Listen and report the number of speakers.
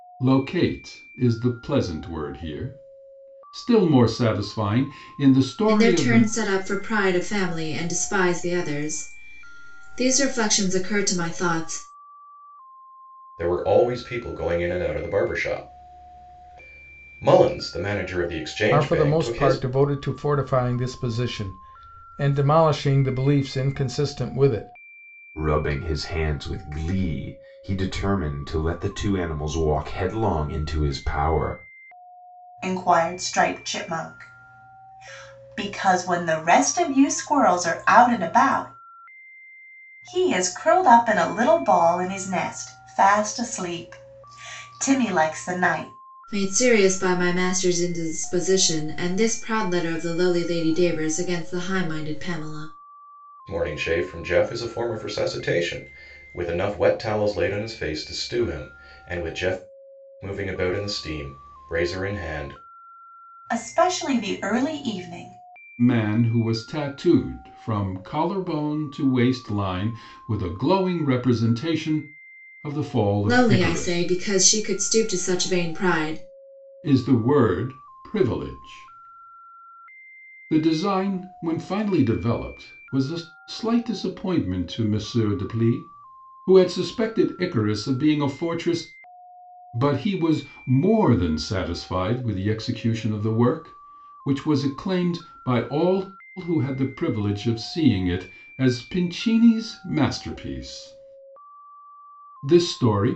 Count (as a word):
six